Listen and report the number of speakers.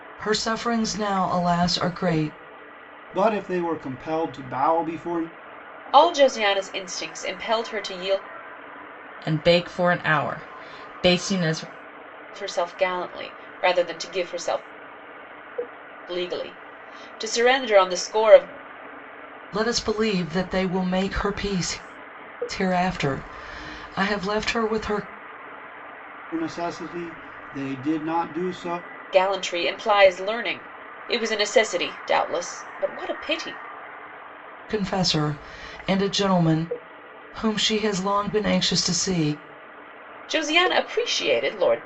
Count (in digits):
4